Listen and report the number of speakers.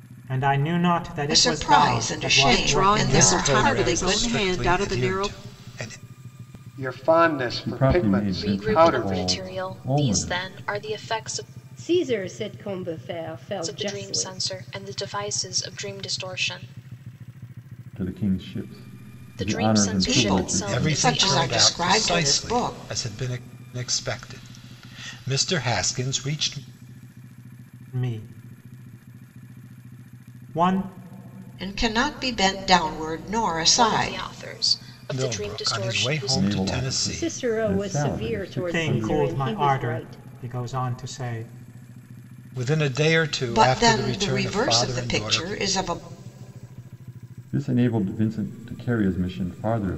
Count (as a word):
eight